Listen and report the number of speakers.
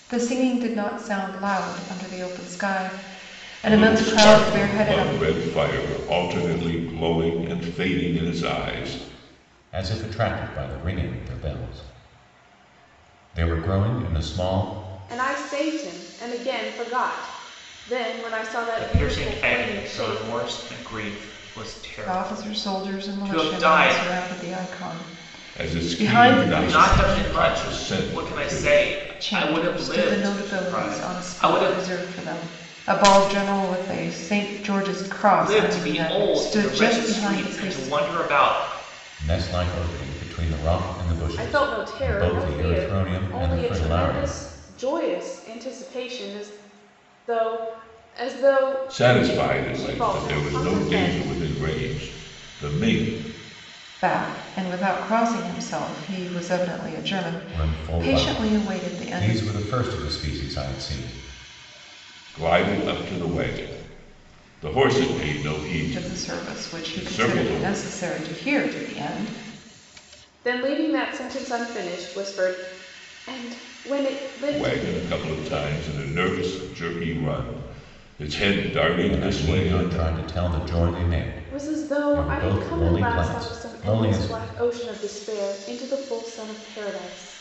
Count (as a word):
five